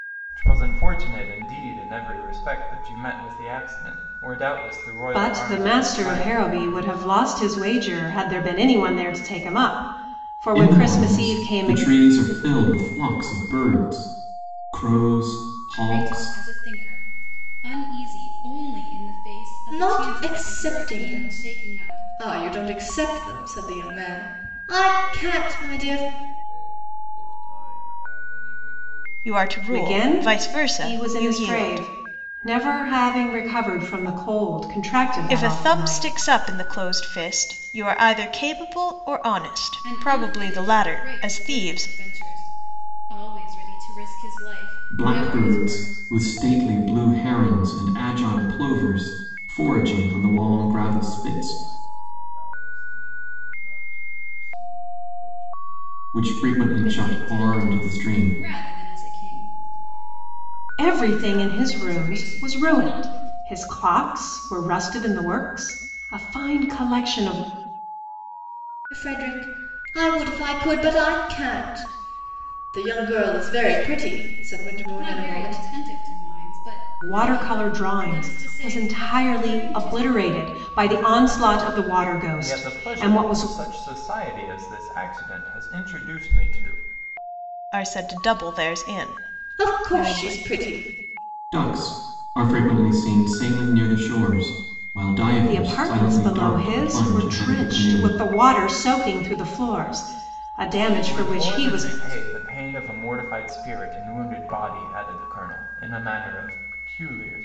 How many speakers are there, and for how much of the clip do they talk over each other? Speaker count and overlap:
7, about 32%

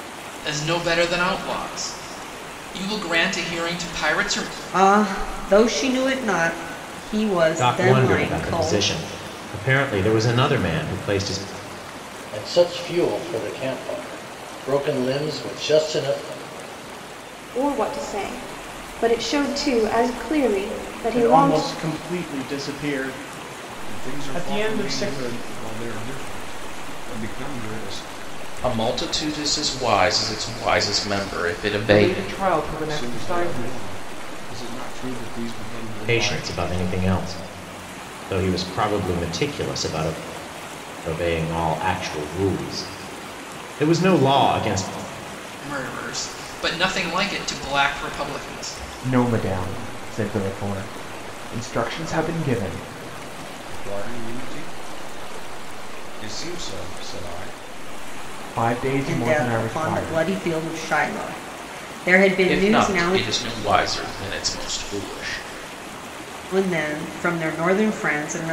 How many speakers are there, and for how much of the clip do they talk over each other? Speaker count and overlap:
9, about 11%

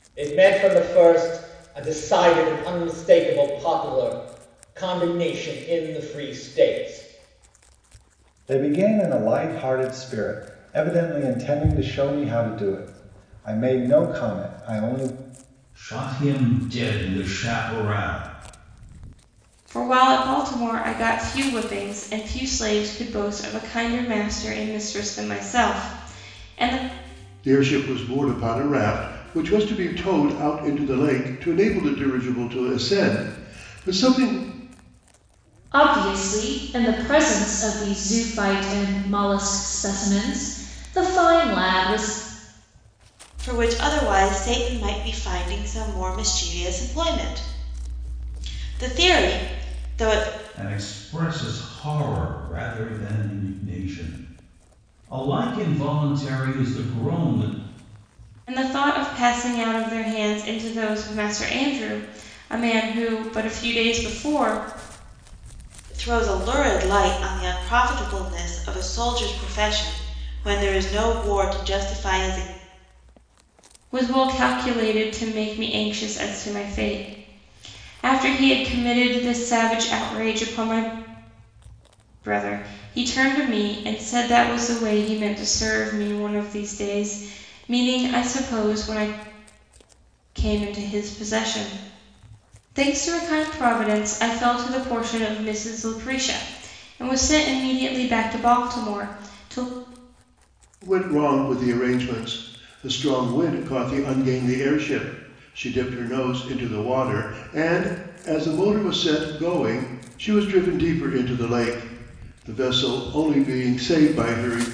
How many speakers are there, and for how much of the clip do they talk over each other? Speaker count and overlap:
7, no overlap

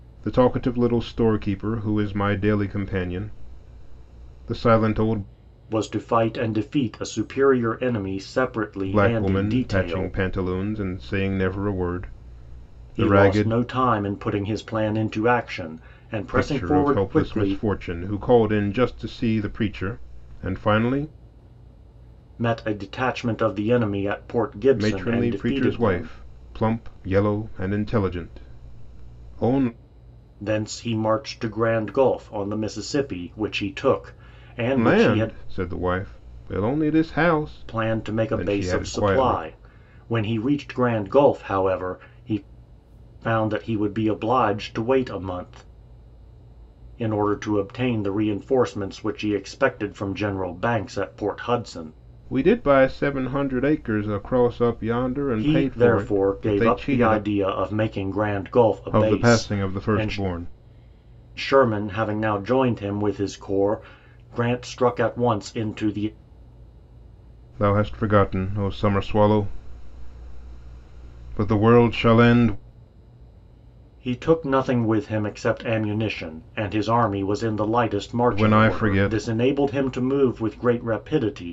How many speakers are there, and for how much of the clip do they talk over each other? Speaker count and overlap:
2, about 14%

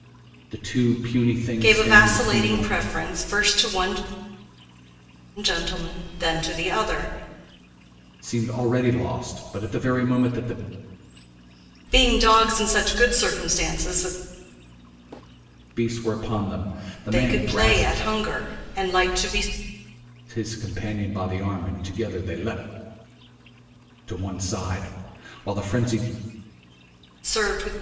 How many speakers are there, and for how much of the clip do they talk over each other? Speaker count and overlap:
2, about 8%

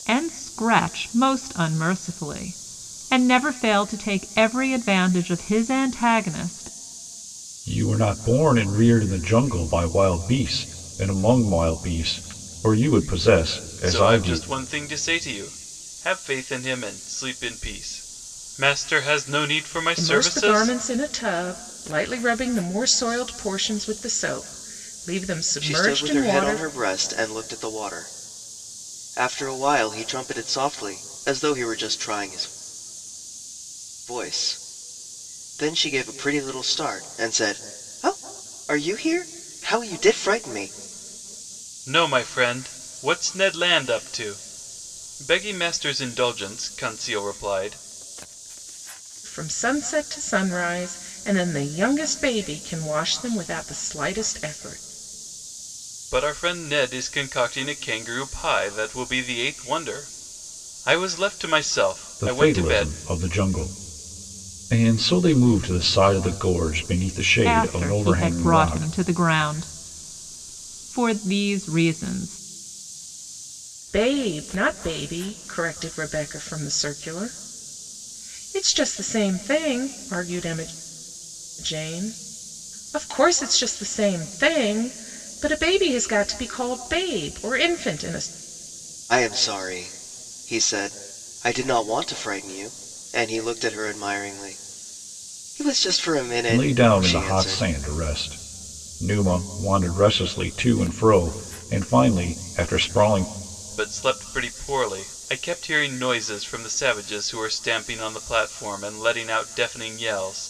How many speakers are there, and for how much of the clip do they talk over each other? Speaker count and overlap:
5, about 5%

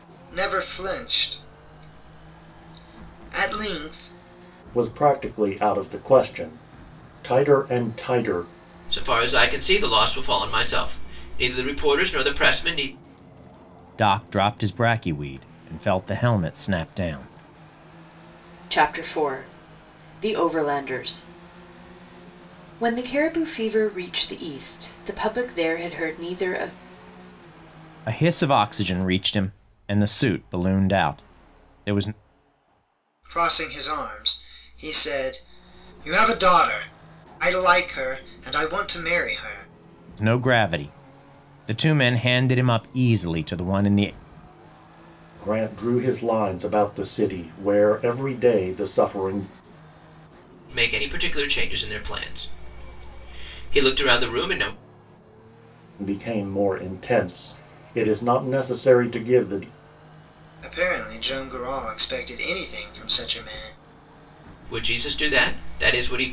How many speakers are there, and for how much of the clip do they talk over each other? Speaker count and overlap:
5, no overlap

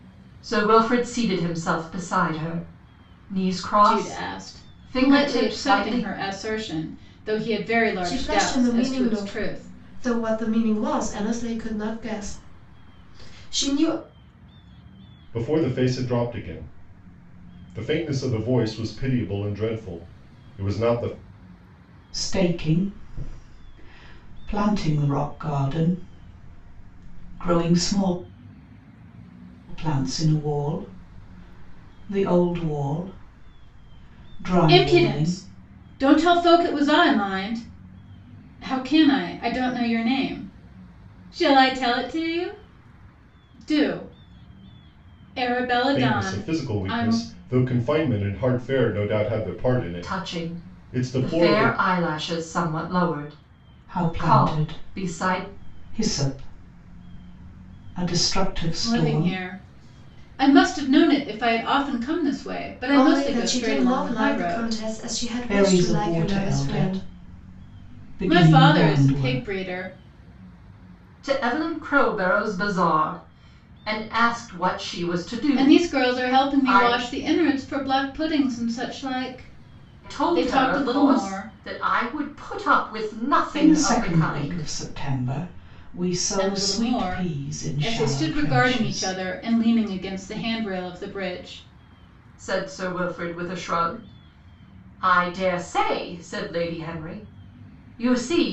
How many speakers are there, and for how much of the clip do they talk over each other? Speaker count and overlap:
5, about 22%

